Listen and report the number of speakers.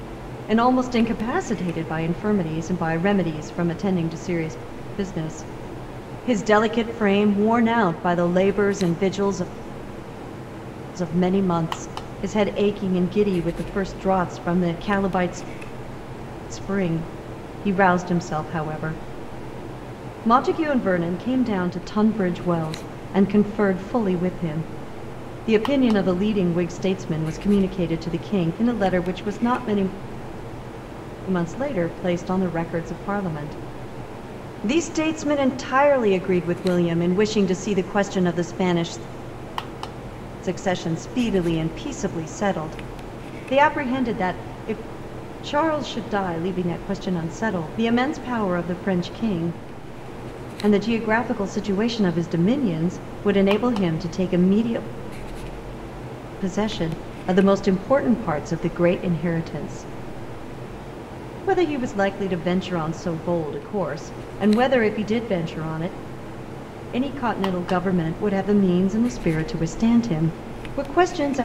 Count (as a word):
one